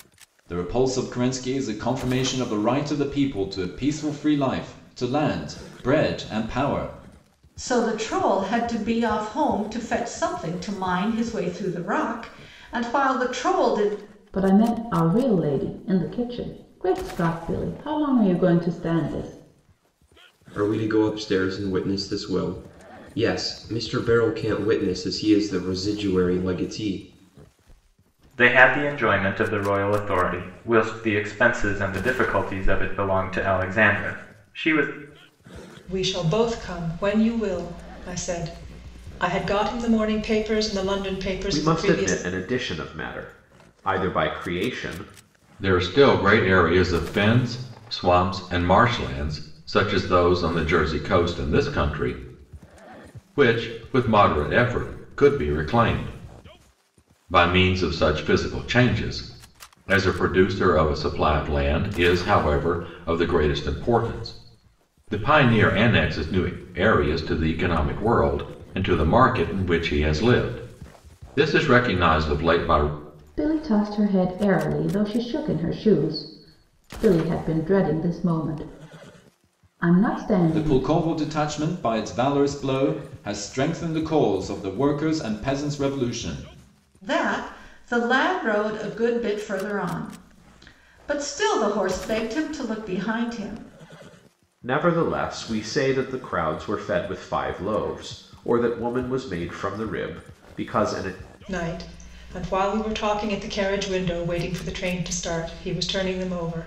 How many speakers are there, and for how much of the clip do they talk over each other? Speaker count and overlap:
eight, about 1%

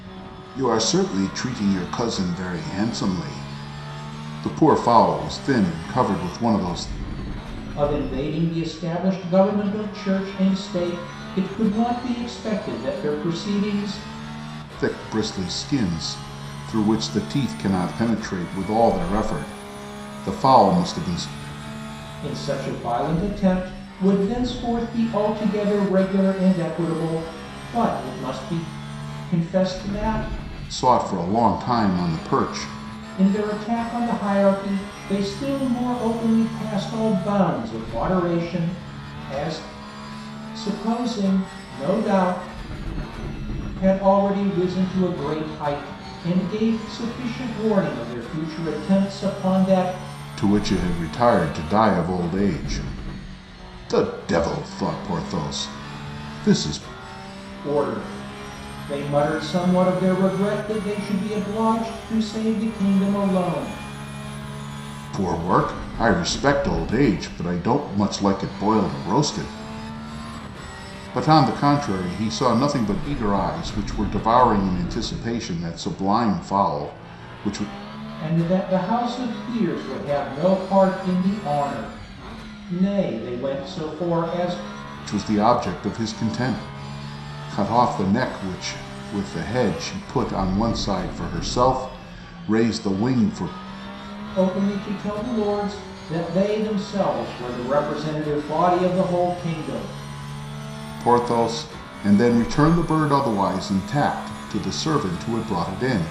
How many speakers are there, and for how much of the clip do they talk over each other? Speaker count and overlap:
two, no overlap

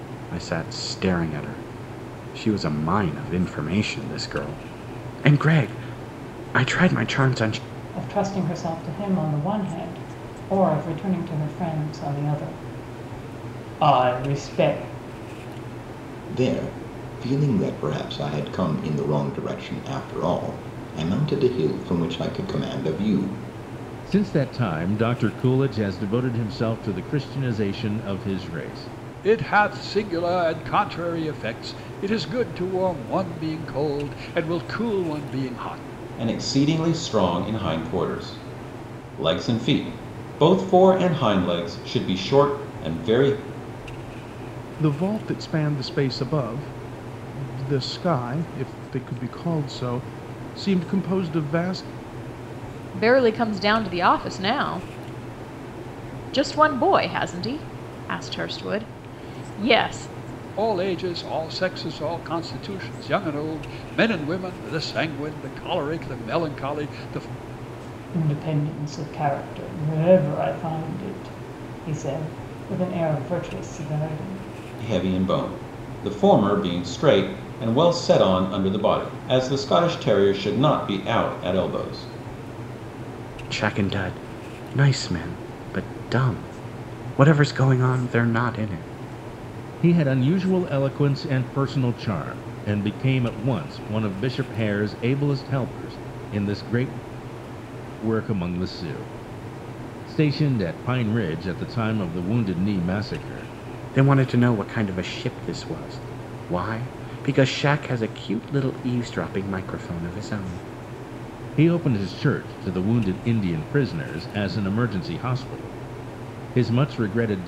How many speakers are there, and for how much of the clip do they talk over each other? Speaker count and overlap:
eight, no overlap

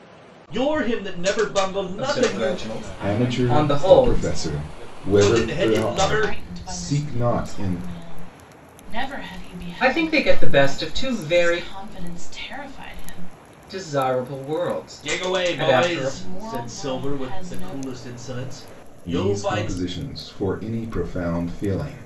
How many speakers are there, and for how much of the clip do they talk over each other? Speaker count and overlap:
five, about 56%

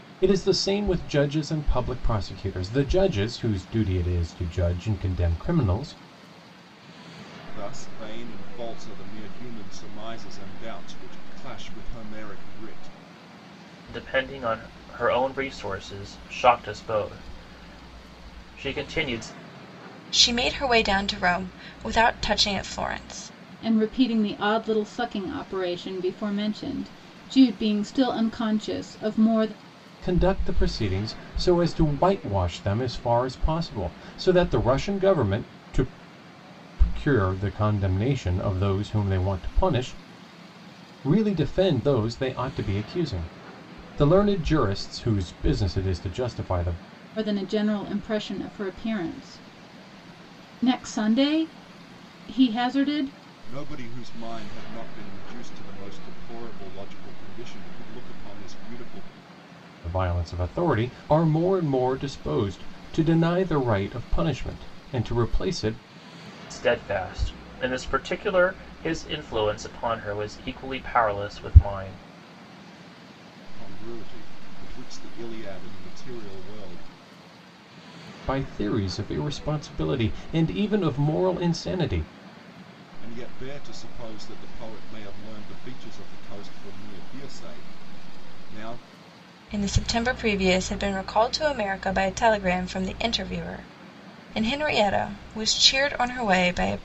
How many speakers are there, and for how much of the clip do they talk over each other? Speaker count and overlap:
five, no overlap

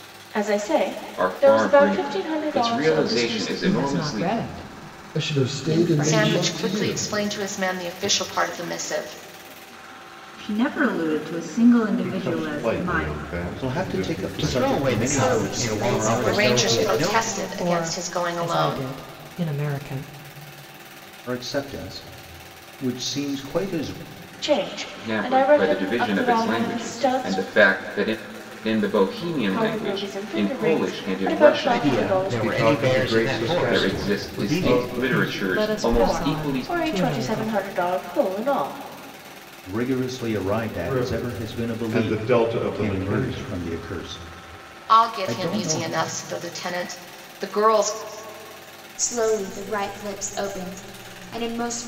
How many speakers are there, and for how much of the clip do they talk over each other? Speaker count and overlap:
ten, about 52%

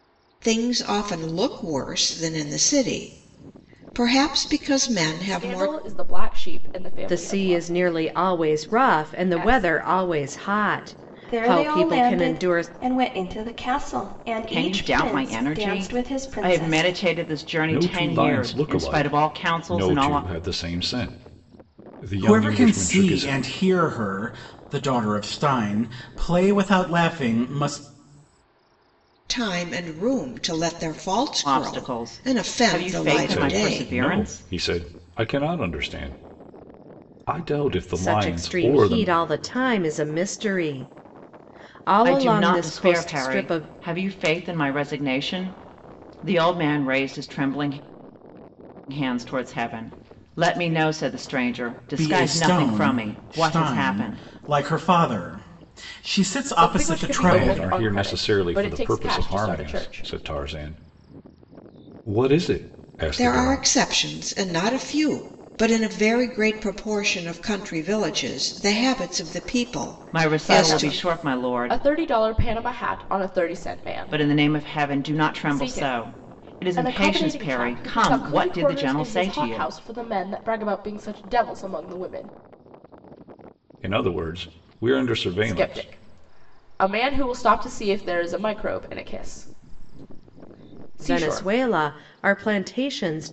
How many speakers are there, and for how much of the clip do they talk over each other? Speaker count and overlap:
seven, about 33%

